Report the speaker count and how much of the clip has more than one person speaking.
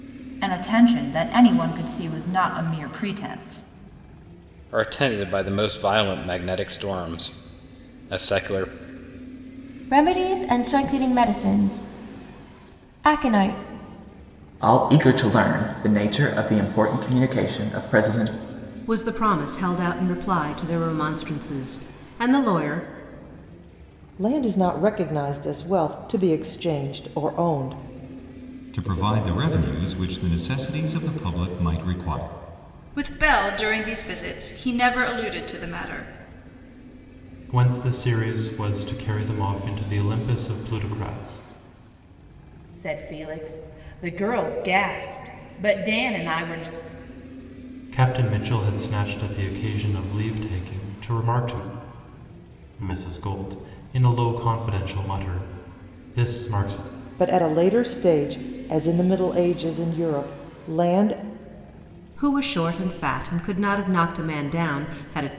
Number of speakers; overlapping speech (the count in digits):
10, no overlap